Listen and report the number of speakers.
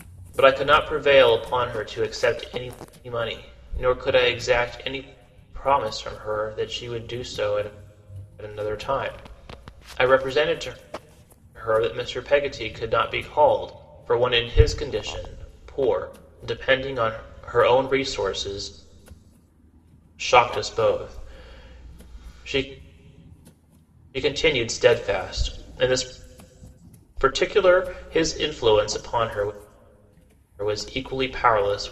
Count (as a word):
one